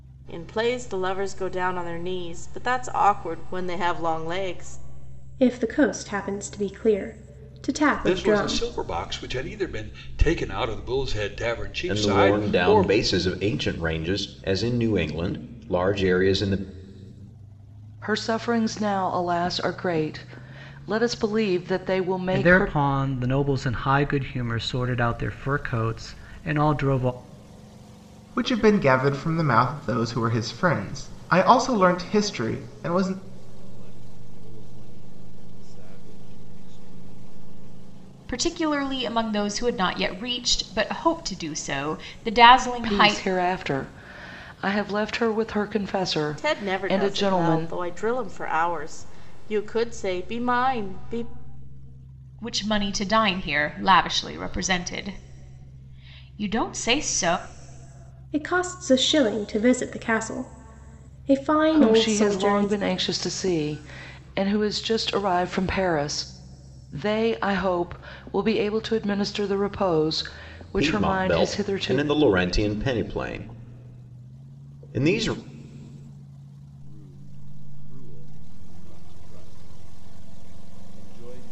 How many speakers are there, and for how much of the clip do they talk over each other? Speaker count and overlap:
9, about 8%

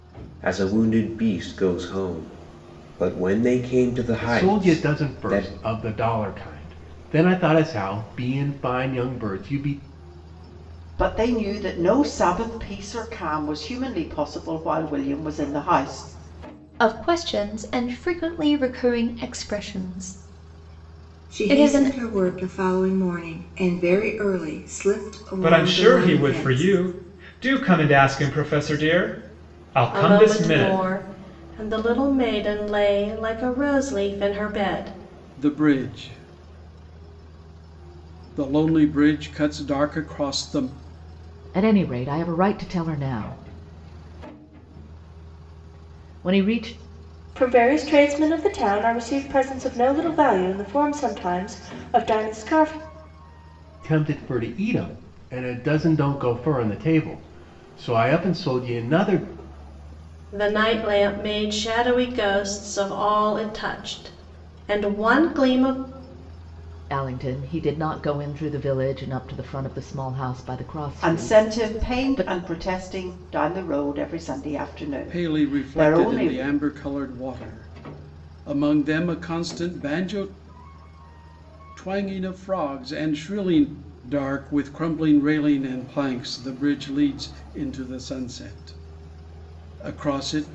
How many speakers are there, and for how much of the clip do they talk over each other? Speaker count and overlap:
10, about 8%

